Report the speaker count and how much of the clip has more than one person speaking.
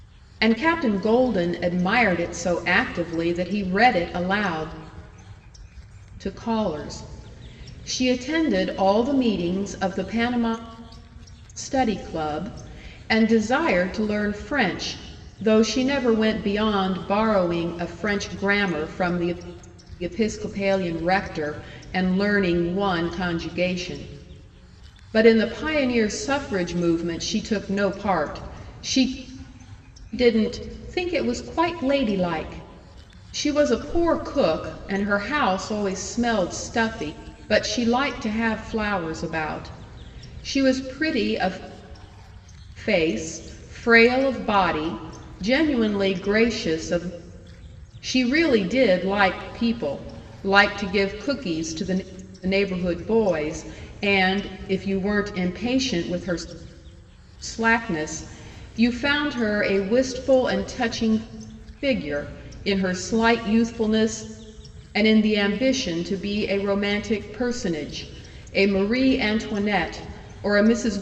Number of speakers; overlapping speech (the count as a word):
one, no overlap